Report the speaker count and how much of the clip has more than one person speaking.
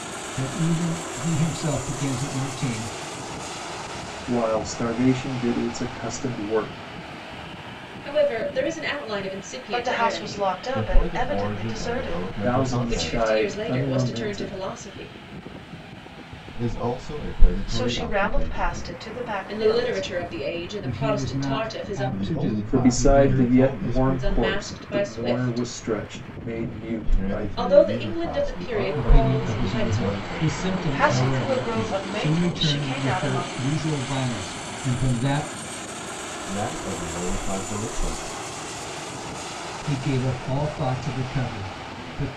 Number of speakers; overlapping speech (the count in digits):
5, about 42%